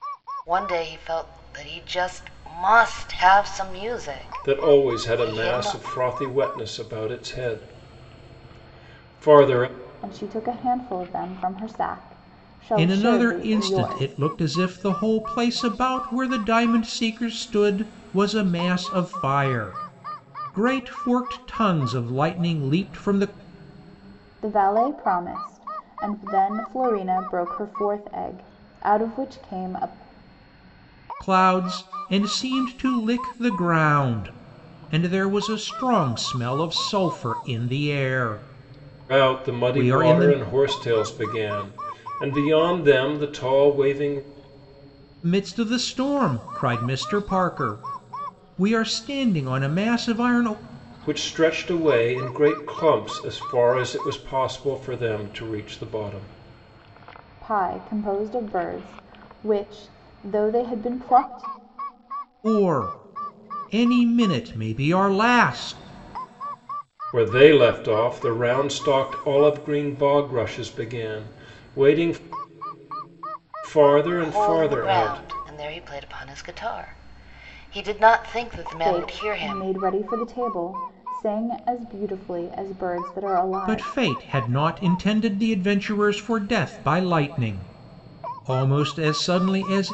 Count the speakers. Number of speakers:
four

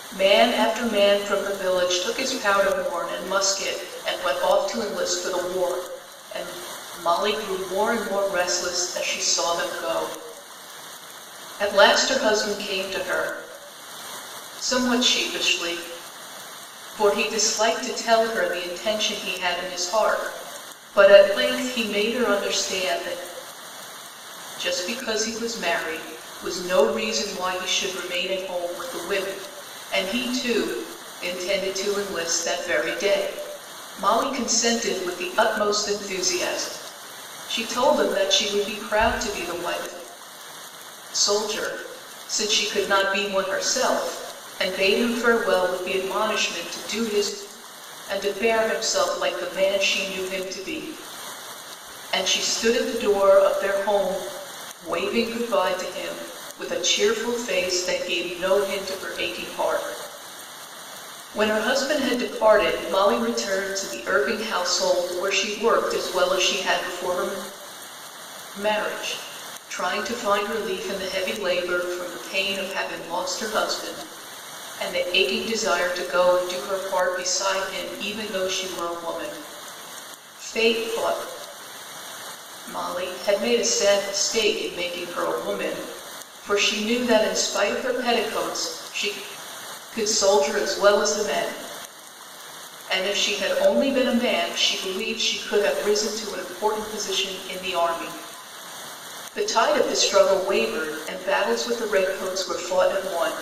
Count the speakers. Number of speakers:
one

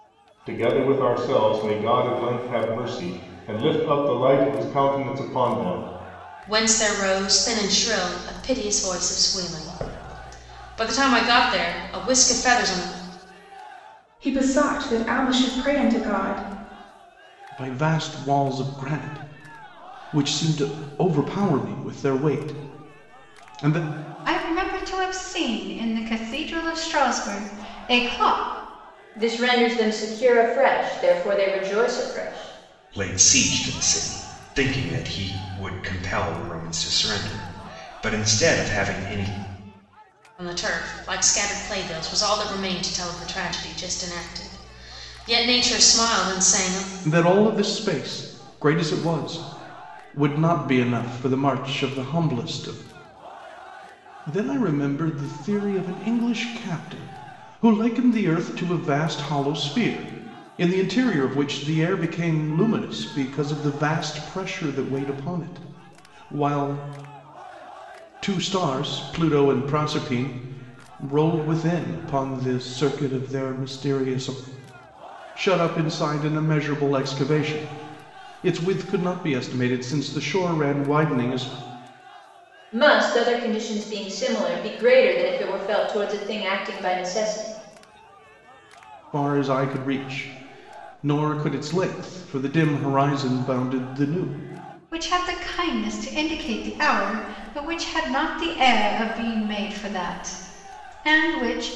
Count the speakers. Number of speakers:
seven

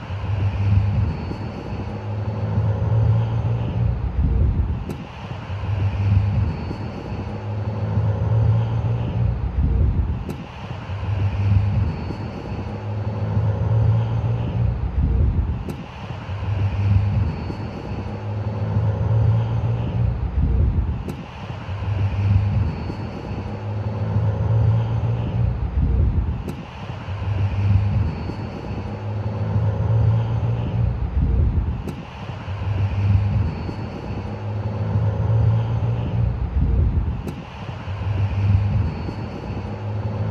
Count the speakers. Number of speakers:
zero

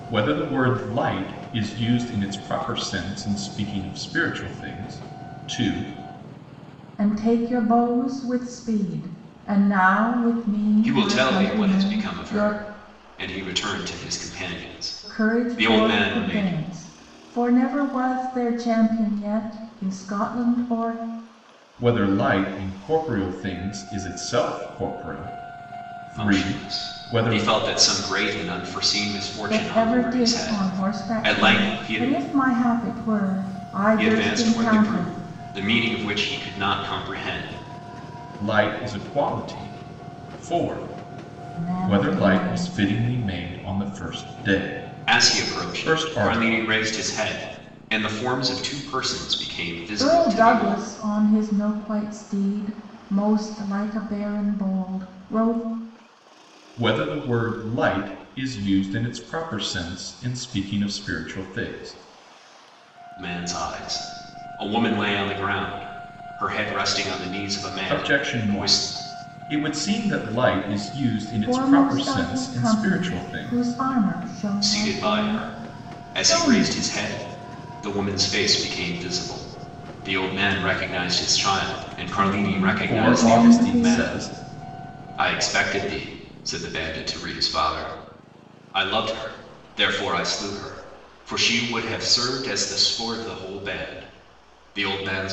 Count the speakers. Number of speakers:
three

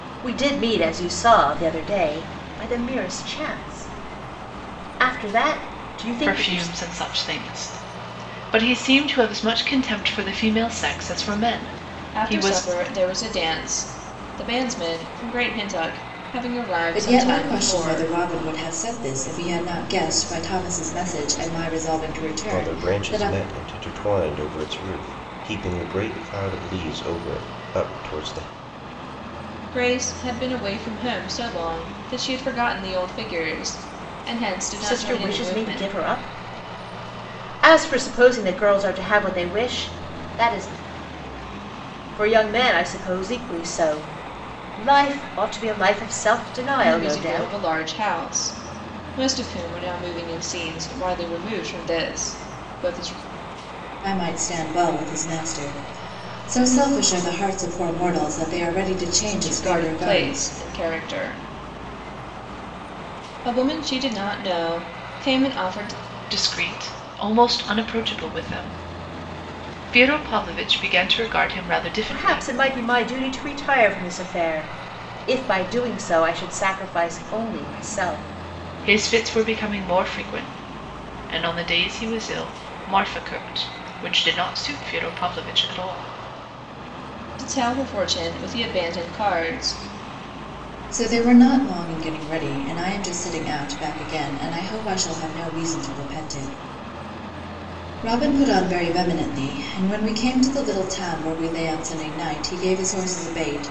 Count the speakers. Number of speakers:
five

